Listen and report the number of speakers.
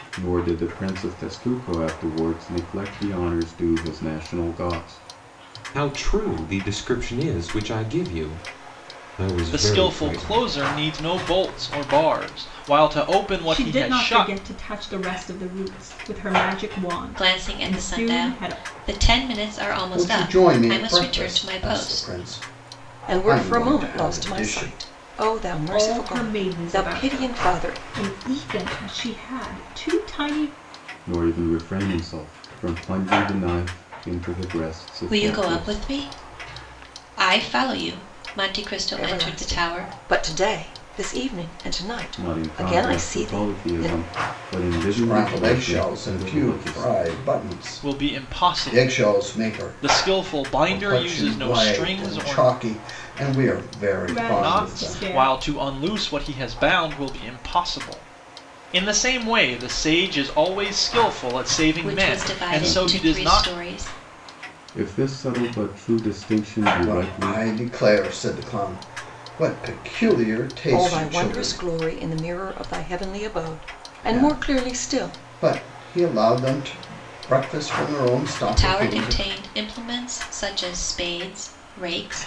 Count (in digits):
7